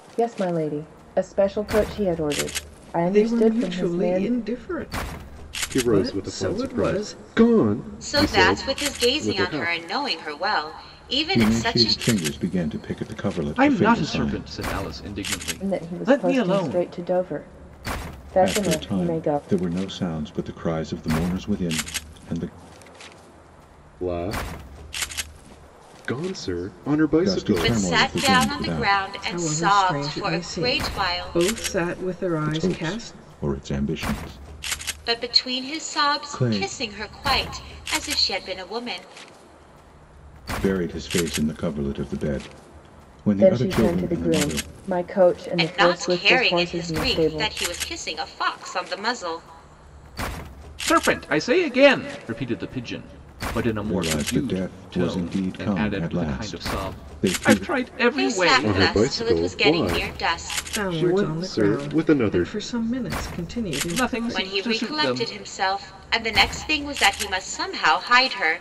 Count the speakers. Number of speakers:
six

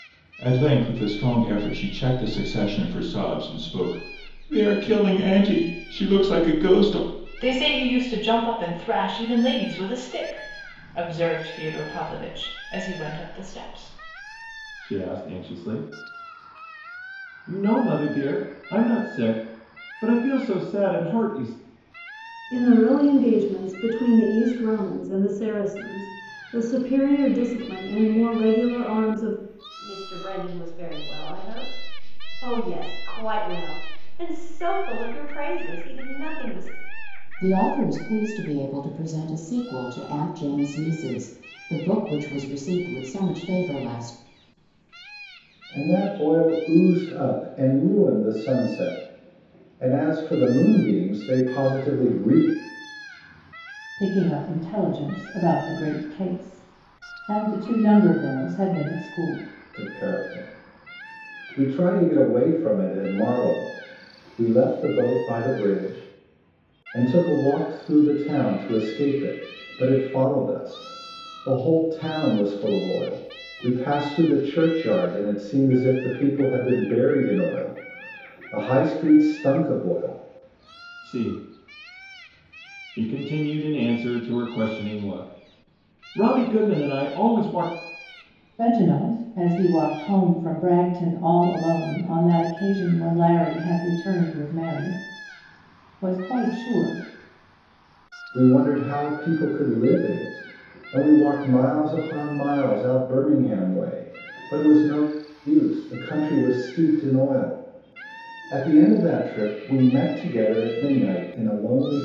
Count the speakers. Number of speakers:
eight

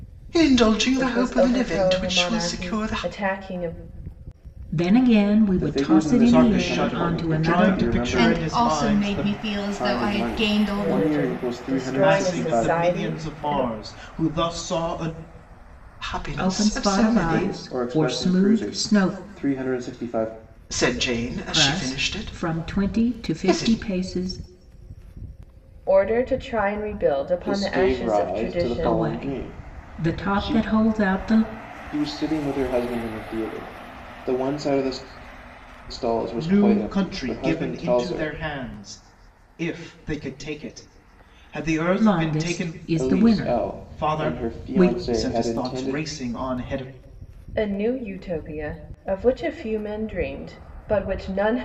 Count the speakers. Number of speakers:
six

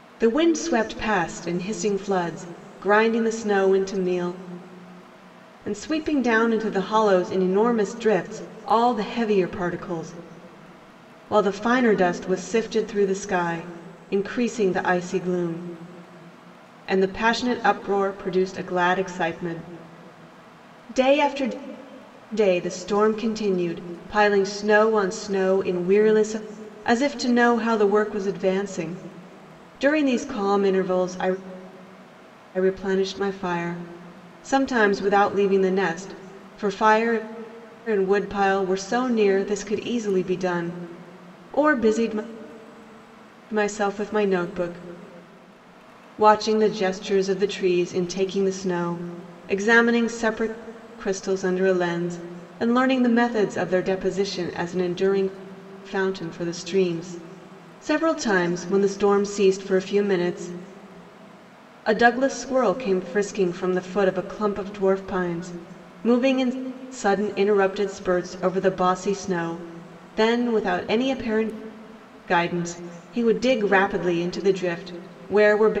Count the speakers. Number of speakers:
one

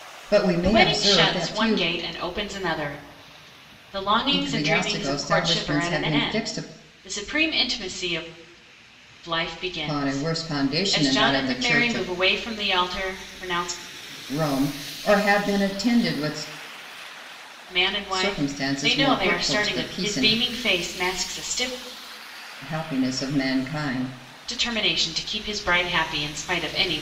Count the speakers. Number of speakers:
two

